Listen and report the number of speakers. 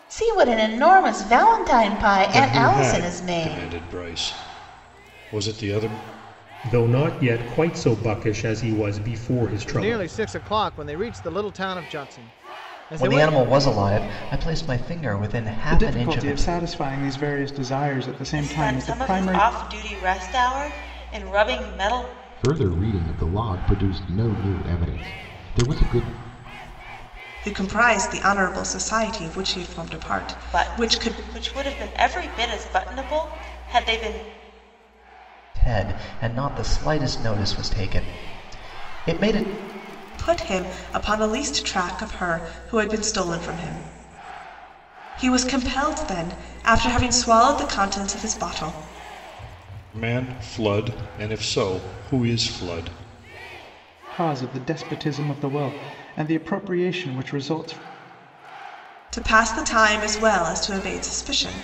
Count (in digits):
9